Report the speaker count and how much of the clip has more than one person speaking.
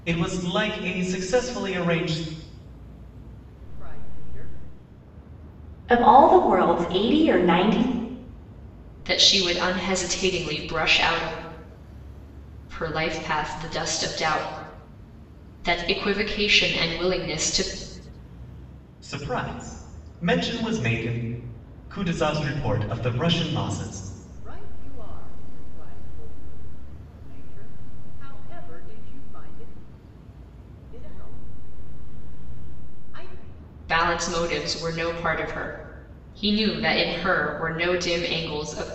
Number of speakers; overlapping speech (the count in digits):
4, no overlap